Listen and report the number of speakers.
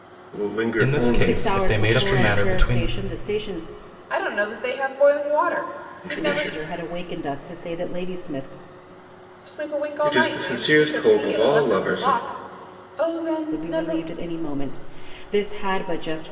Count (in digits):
4